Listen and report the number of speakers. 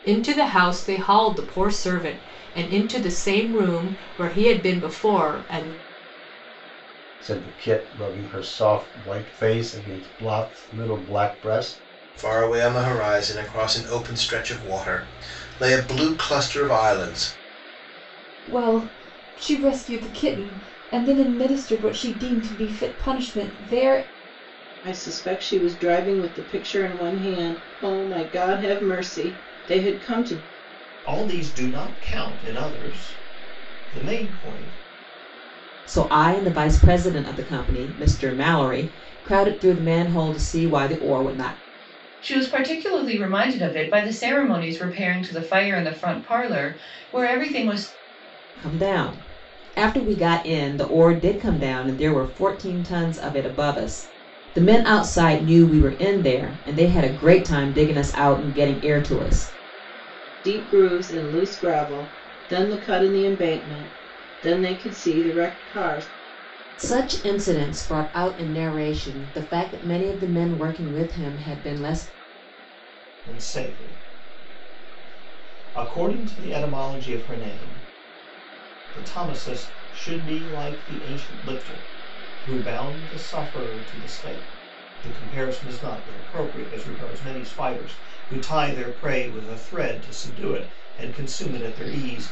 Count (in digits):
8